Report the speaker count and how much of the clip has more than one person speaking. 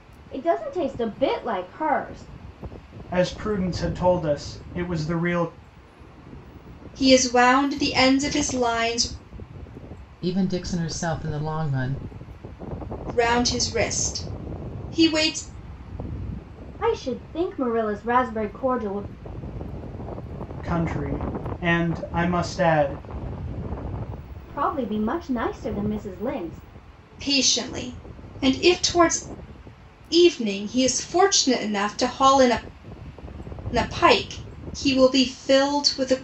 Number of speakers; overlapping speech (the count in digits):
4, no overlap